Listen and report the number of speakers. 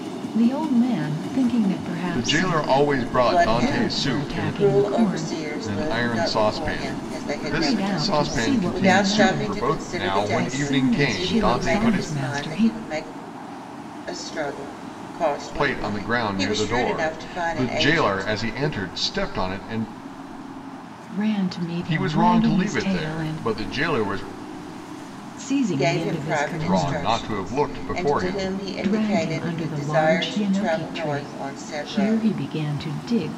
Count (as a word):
three